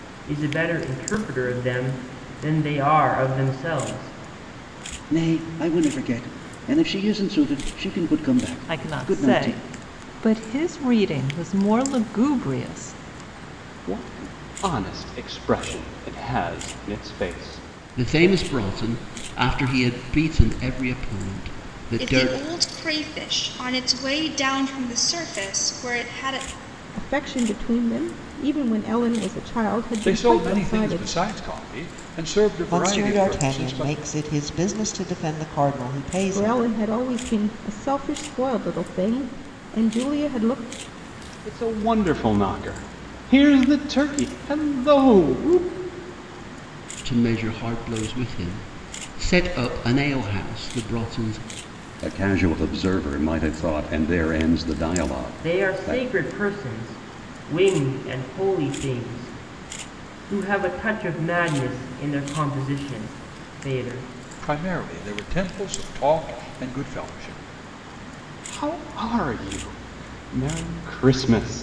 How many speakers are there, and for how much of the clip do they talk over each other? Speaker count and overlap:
nine, about 7%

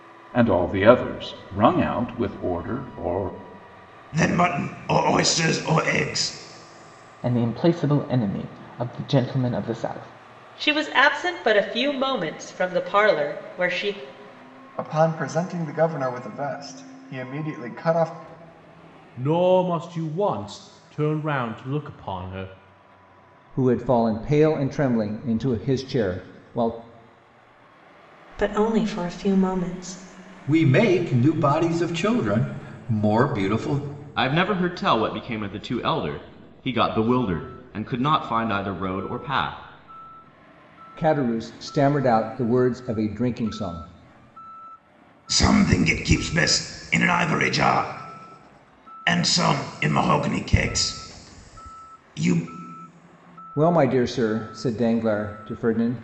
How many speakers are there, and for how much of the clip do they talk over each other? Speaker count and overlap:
ten, no overlap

